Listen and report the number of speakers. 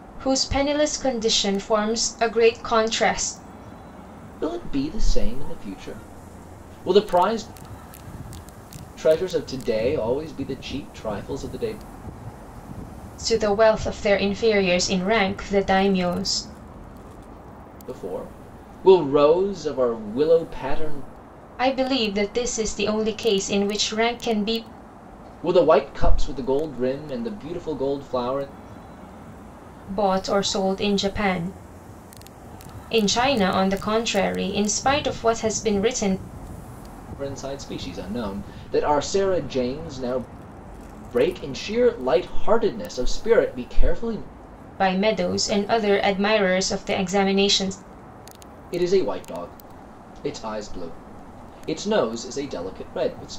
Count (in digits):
2